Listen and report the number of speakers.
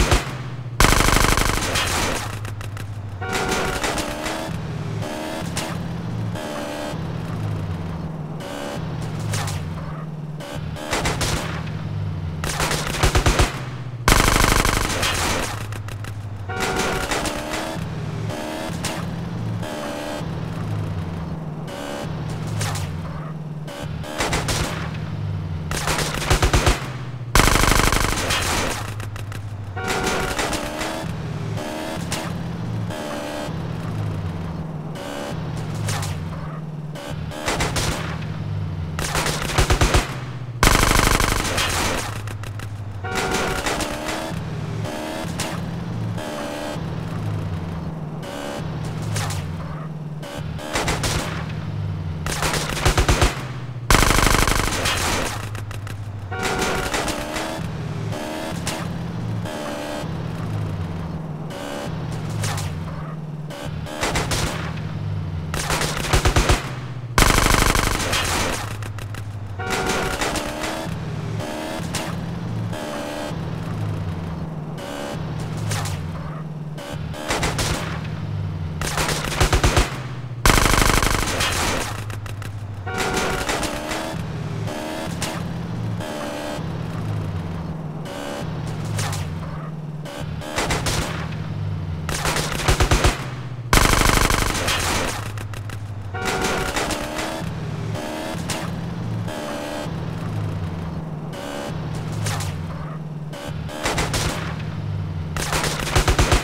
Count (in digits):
0